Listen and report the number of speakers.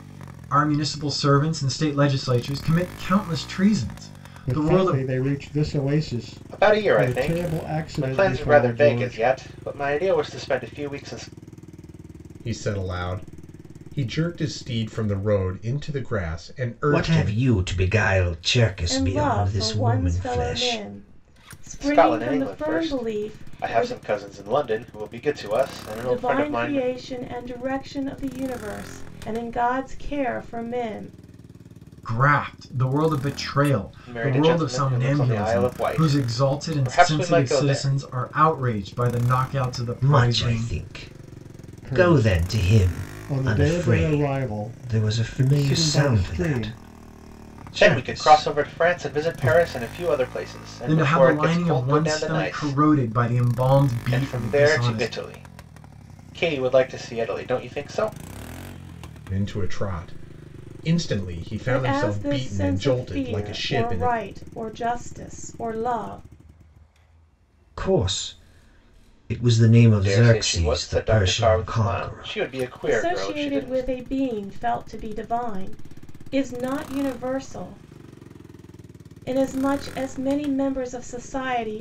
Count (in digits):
6